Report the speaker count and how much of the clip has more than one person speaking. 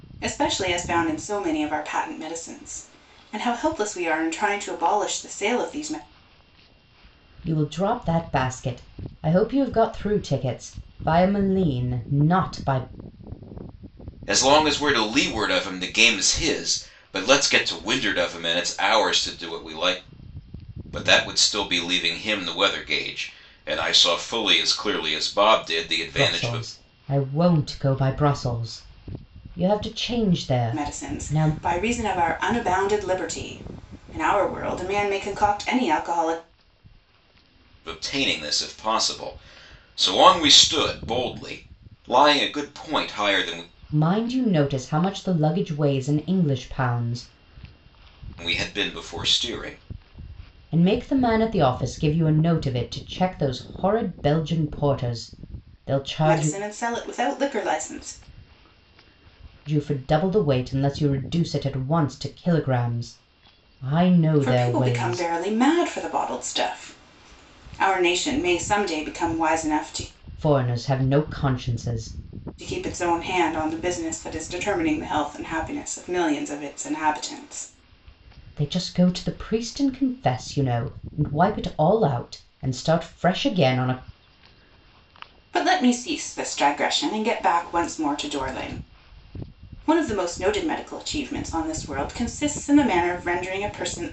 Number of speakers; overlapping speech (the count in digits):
3, about 3%